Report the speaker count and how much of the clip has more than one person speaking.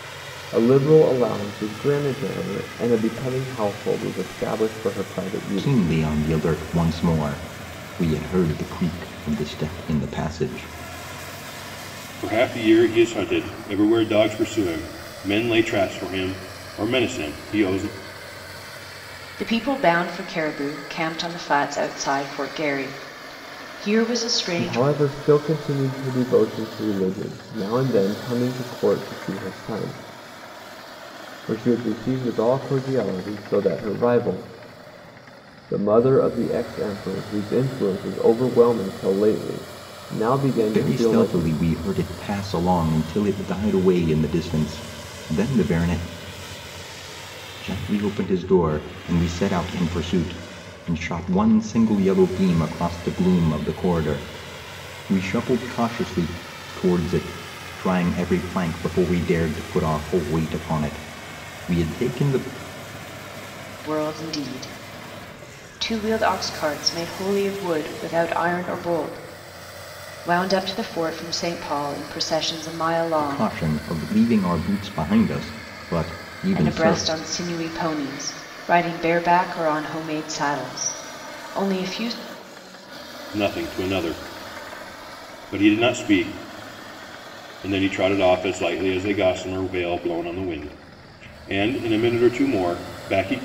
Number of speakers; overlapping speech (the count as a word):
four, about 3%